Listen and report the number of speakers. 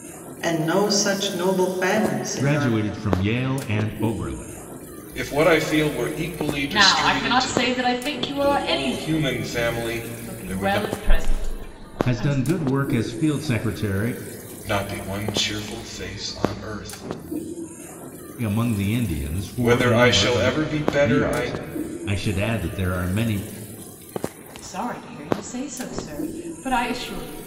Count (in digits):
4